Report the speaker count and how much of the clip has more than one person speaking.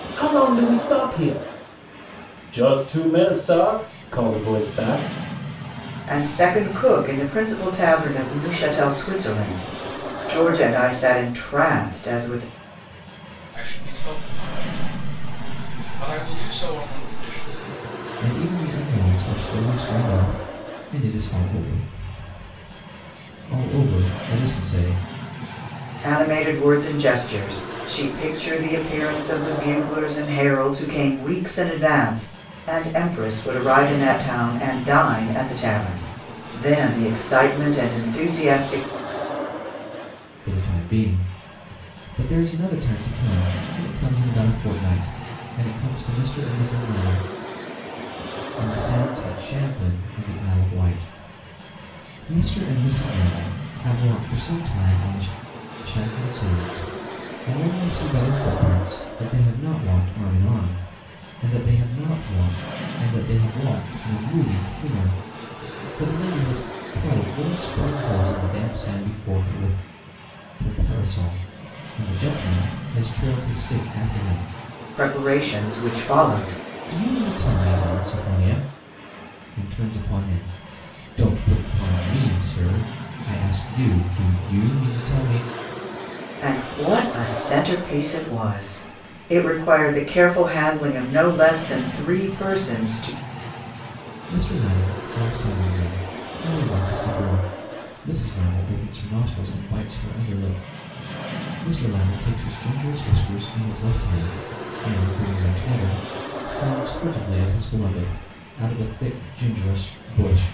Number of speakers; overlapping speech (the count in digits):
4, no overlap